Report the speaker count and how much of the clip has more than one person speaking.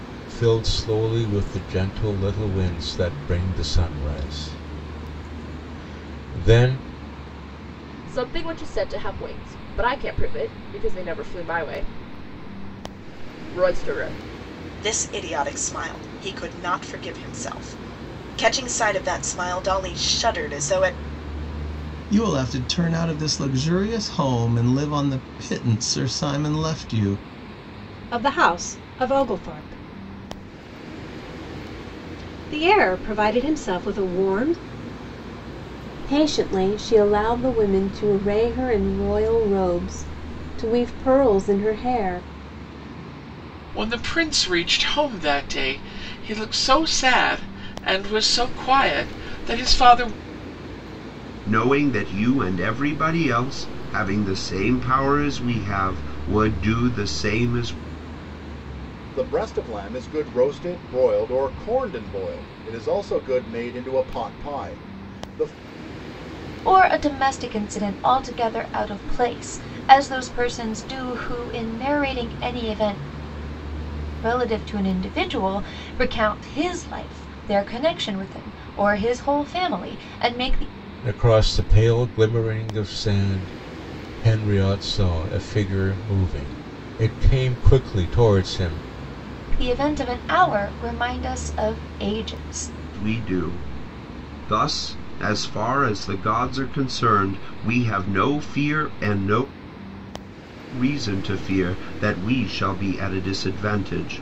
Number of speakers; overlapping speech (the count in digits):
10, no overlap